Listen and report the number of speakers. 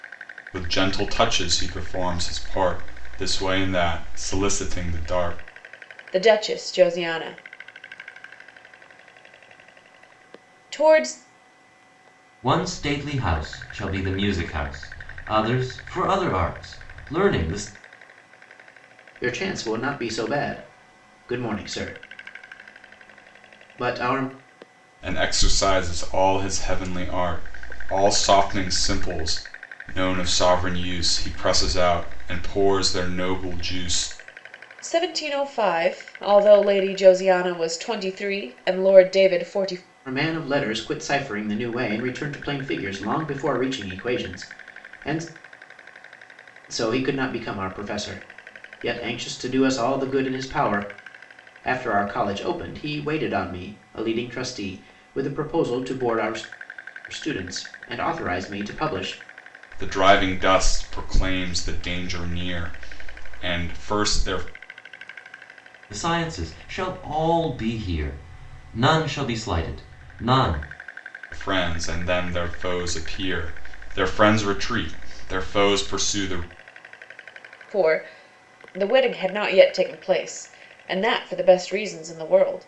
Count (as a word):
four